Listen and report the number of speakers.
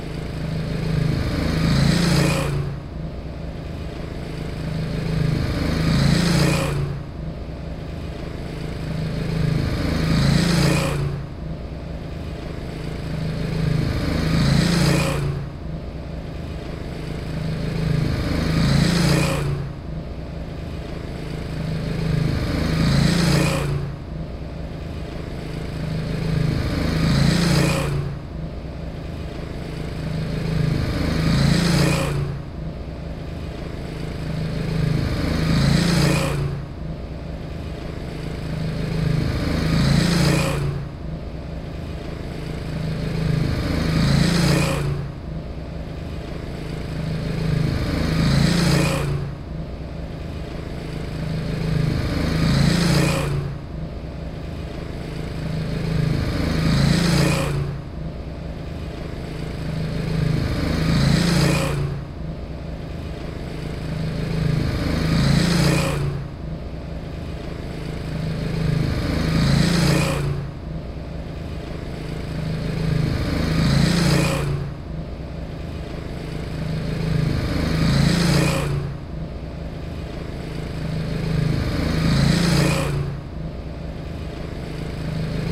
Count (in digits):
0